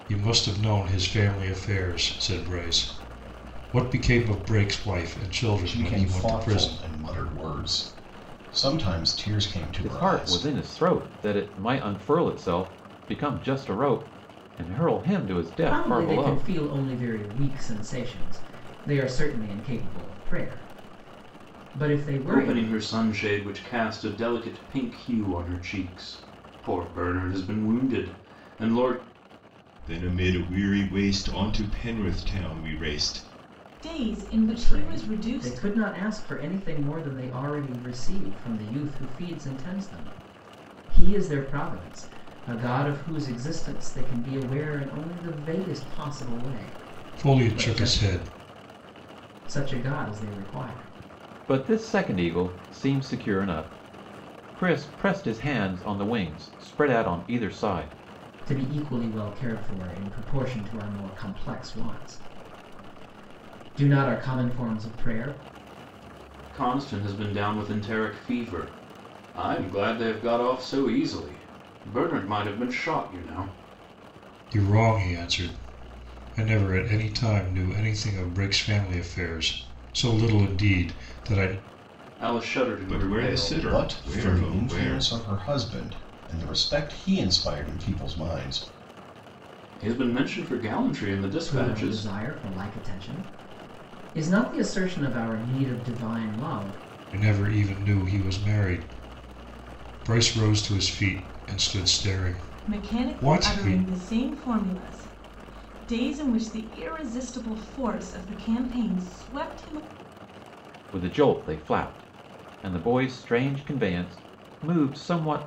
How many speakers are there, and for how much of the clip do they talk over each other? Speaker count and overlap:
7, about 8%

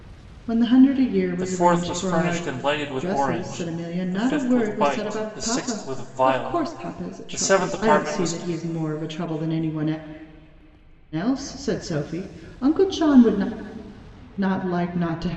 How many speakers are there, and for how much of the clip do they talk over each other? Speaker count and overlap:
2, about 41%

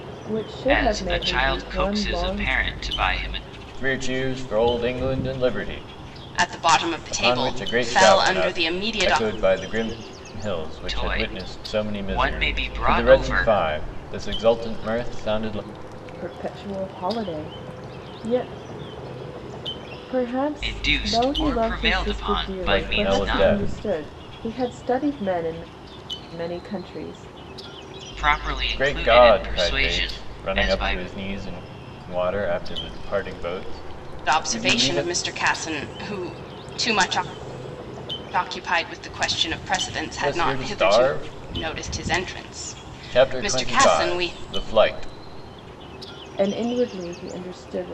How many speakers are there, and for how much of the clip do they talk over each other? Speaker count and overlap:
4, about 32%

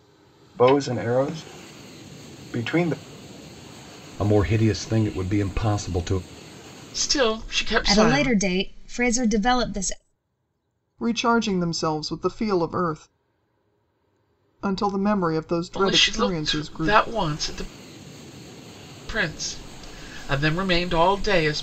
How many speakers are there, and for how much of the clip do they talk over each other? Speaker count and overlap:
5, about 9%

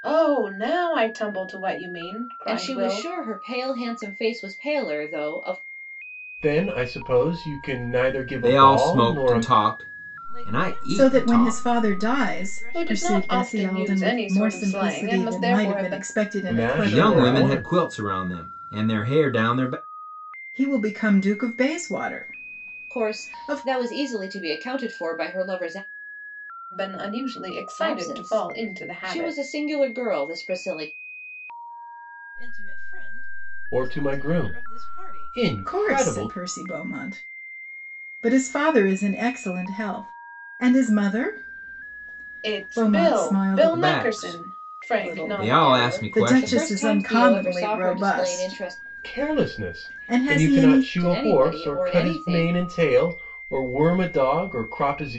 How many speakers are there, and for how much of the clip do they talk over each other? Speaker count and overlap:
6, about 43%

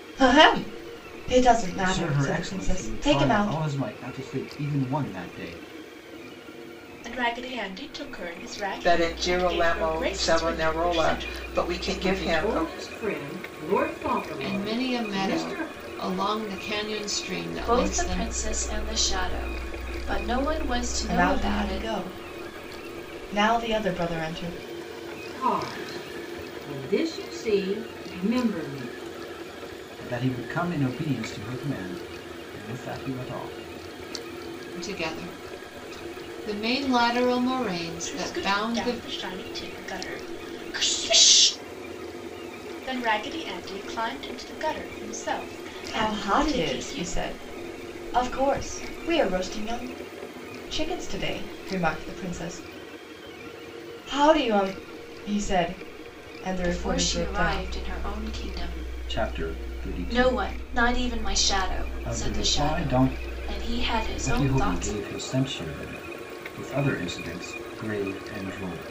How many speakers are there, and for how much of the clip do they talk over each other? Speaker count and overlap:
7, about 24%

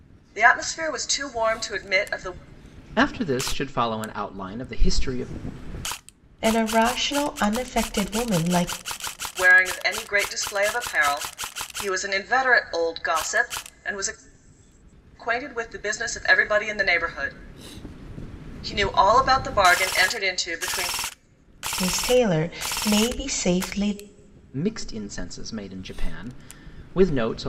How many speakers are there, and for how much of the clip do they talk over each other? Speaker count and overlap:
3, no overlap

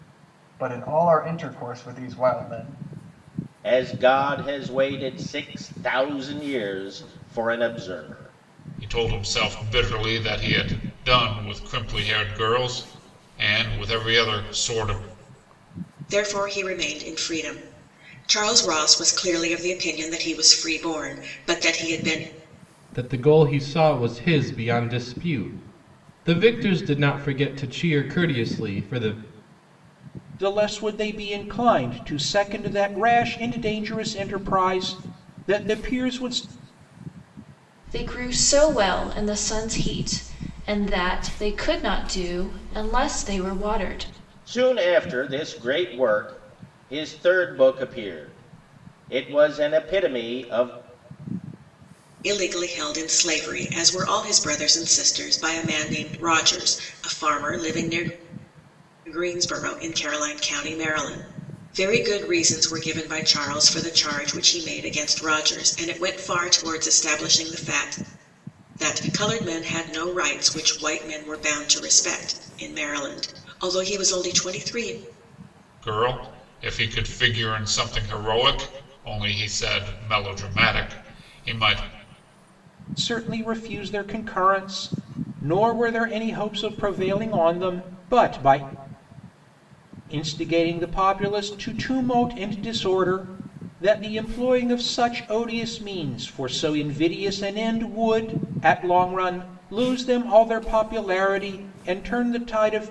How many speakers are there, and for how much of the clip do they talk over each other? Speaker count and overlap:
7, no overlap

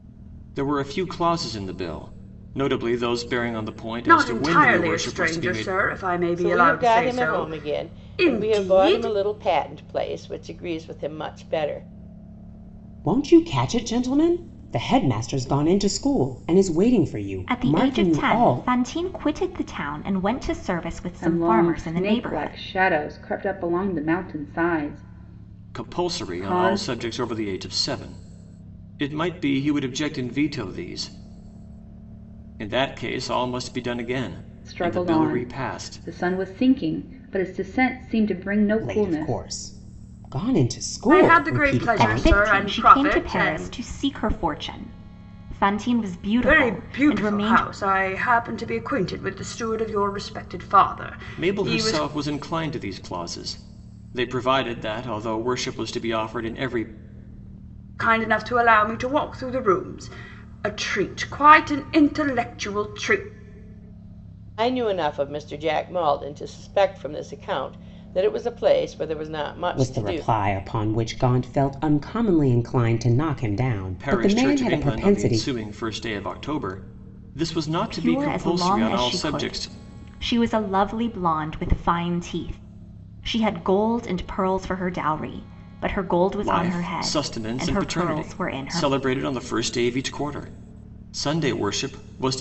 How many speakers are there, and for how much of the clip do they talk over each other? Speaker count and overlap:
6, about 24%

